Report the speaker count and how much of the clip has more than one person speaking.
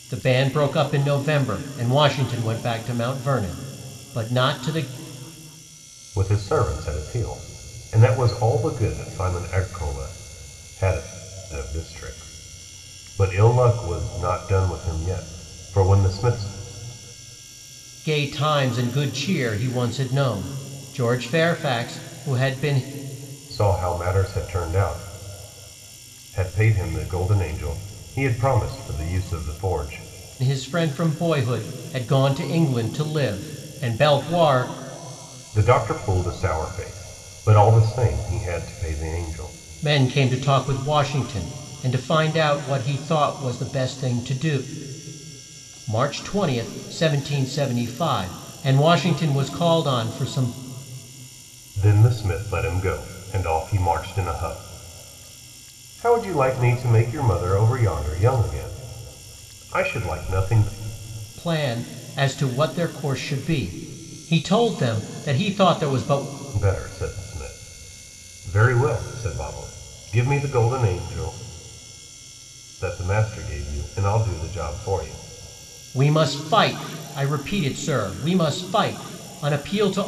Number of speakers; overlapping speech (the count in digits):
2, no overlap